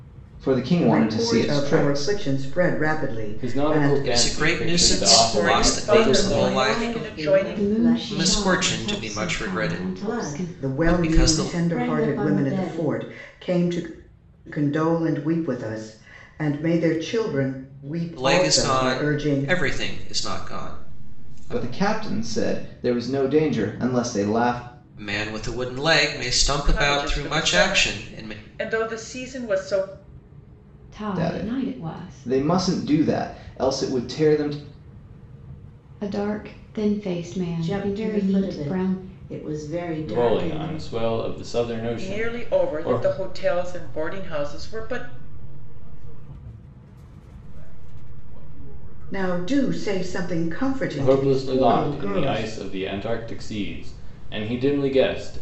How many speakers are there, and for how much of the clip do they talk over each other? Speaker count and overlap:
8, about 51%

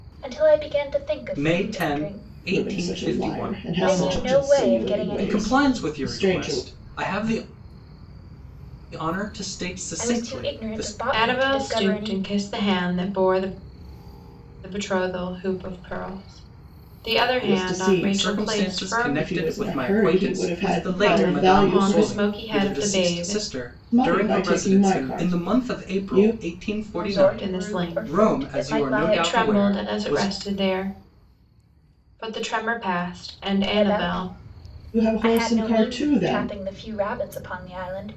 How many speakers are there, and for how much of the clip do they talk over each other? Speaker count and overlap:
4, about 55%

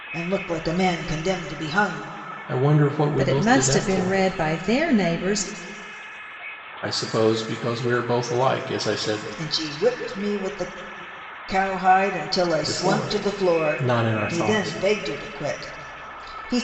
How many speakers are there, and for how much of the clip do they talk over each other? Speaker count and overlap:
3, about 22%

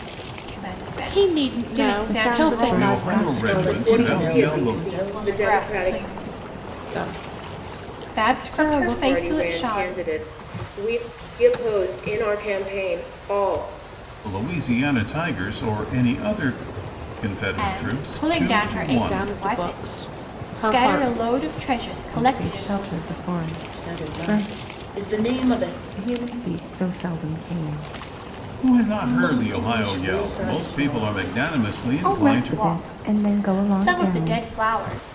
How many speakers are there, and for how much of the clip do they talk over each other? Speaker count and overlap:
6, about 46%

